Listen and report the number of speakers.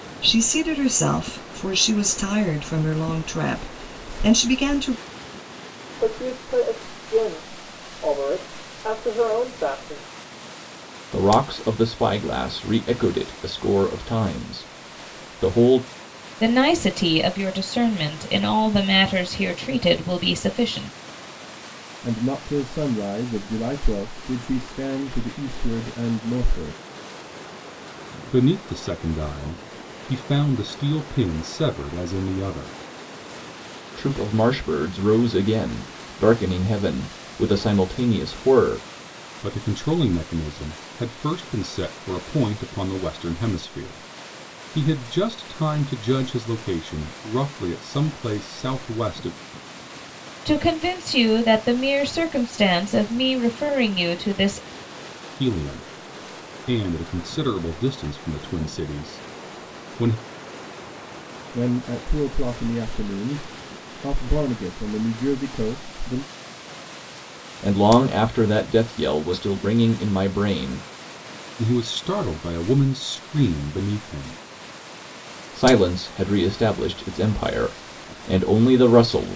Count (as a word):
six